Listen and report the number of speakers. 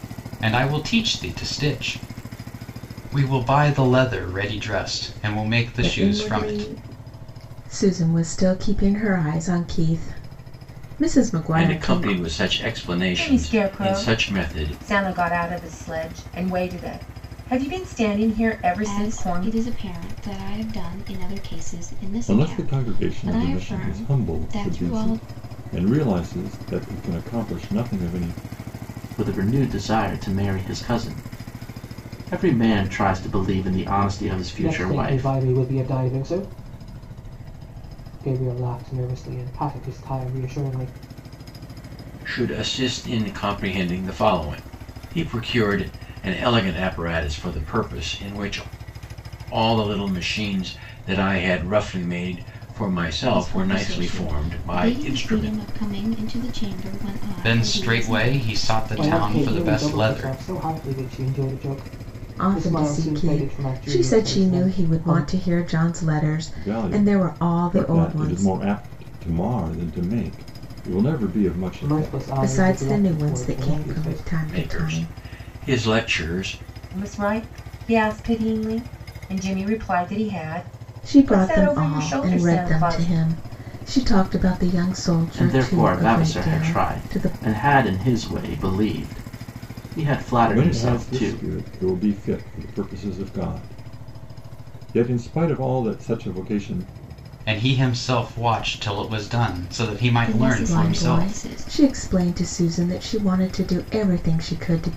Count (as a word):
eight